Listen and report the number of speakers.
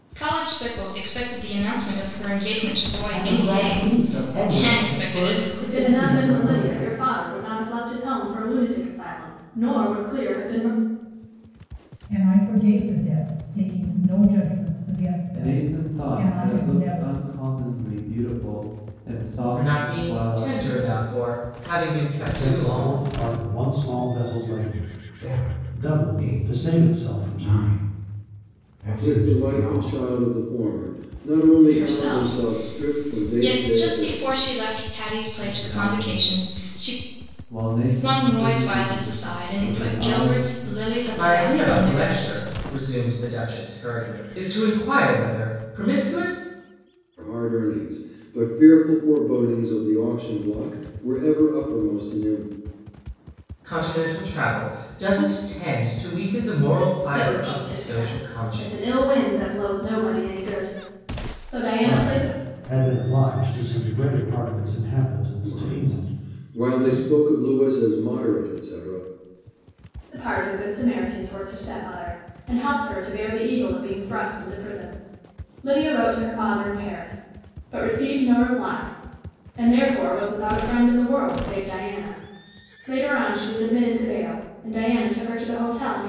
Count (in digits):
9